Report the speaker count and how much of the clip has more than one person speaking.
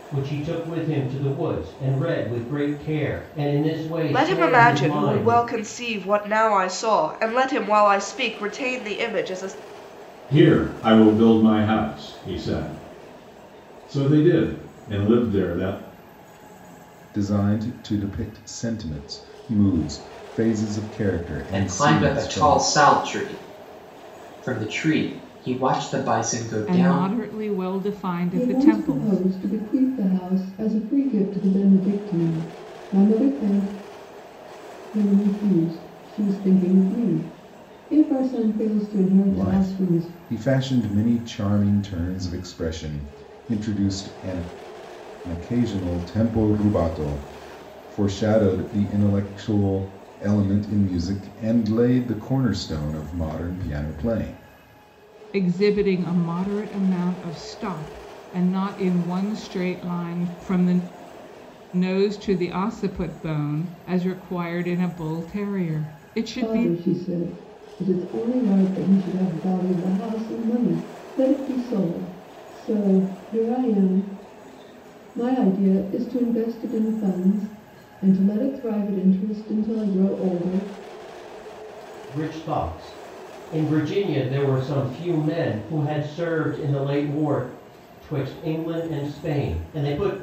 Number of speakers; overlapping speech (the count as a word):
seven, about 6%